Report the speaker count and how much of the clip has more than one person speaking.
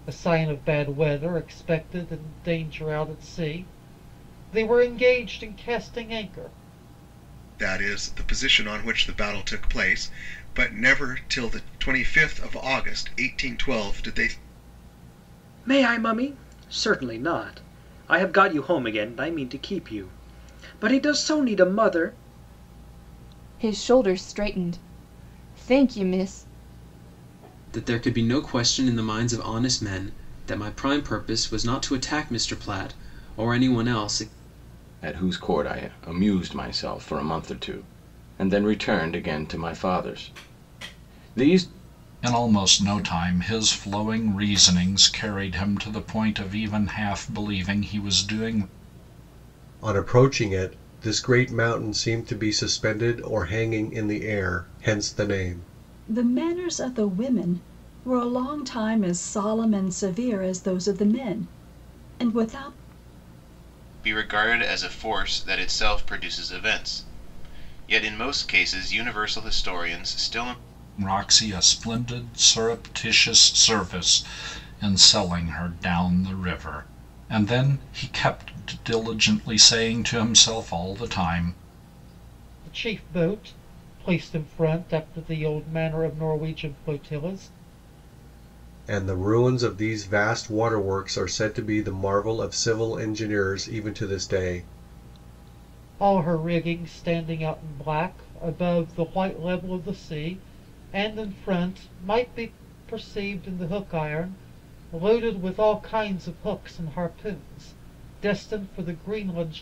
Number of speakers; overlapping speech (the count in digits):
10, no overlap